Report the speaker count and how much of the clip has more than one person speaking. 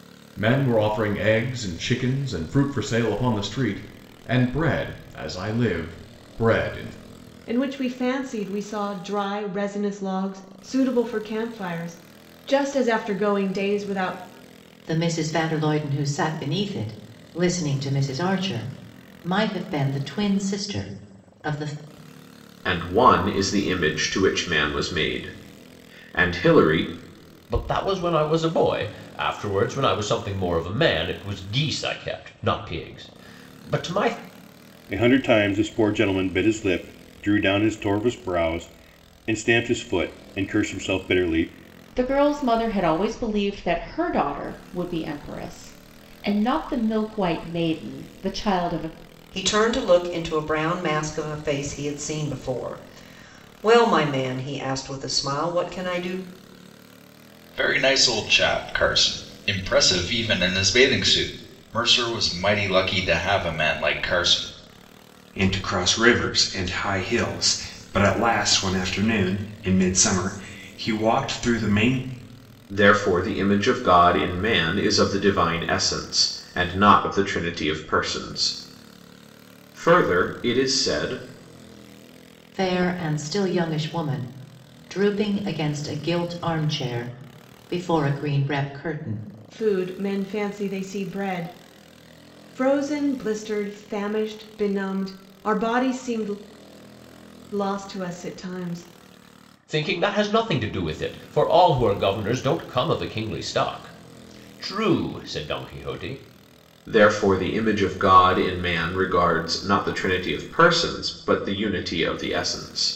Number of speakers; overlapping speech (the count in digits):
10, no overlap